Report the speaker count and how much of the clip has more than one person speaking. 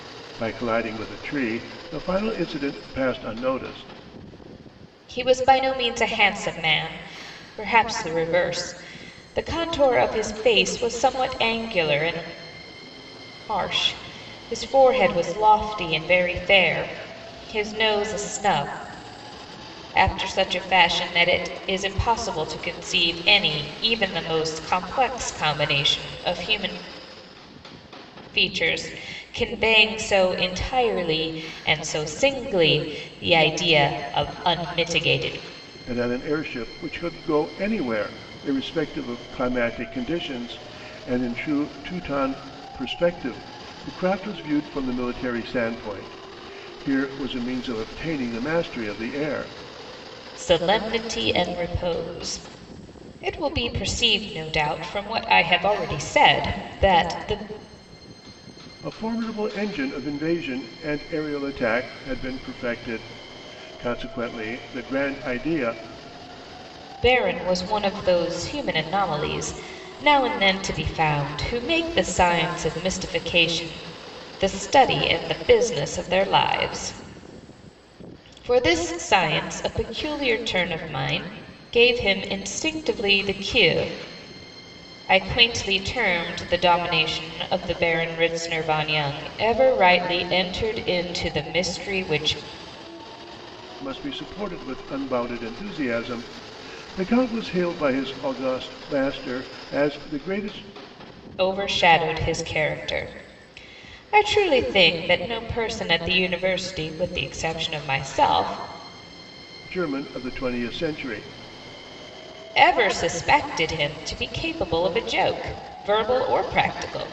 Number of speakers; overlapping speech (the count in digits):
2, no overlap